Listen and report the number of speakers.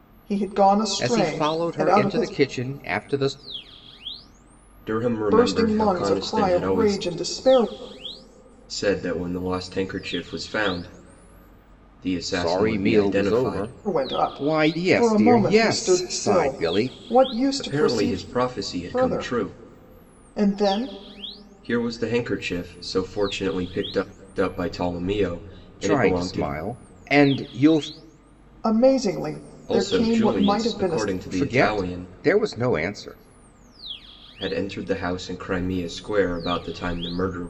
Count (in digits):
3